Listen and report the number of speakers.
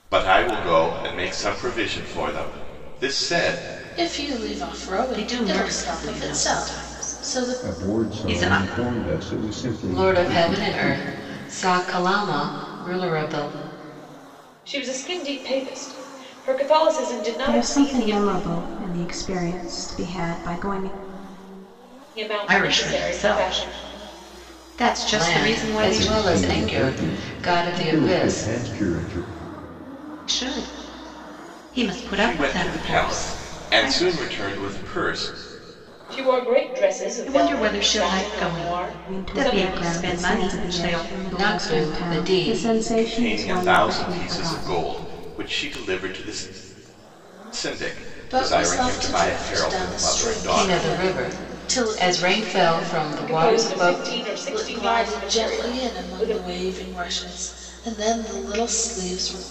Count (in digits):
7